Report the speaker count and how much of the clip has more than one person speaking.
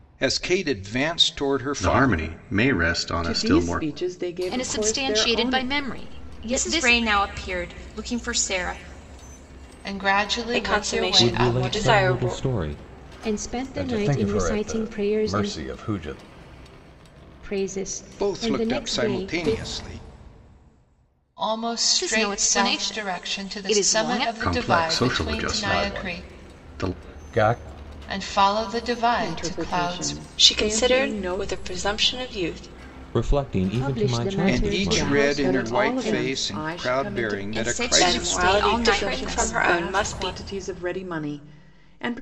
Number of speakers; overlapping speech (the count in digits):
10, about 52%